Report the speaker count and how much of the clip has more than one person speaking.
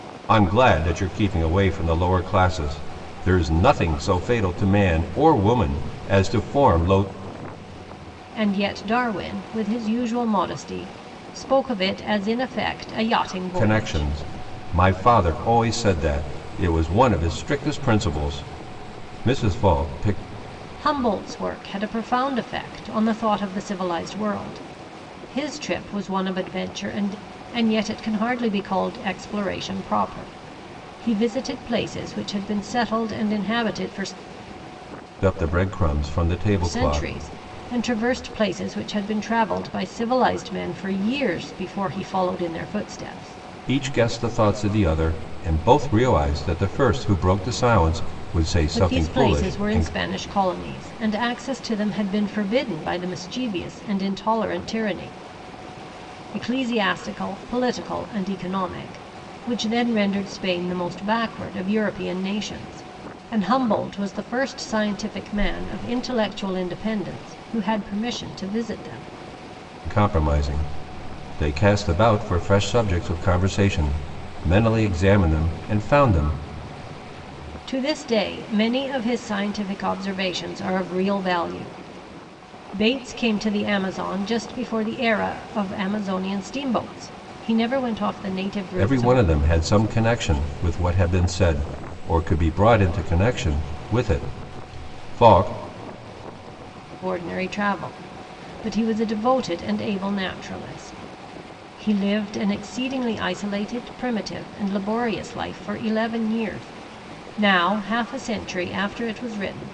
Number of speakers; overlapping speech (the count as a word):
two, about 3%